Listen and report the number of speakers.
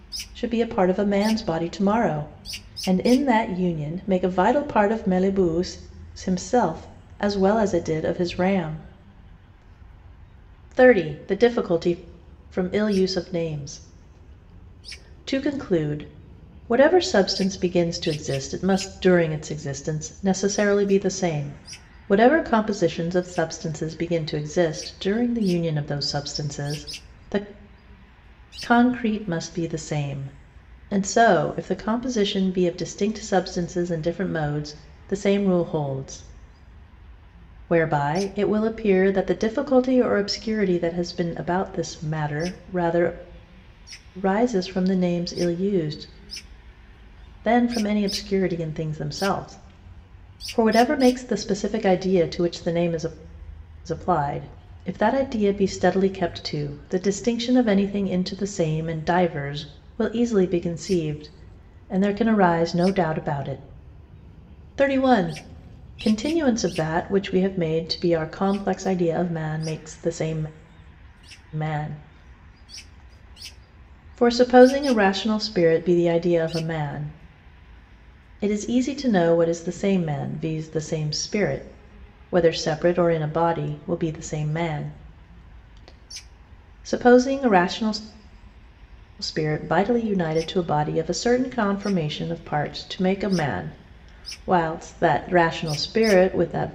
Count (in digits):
1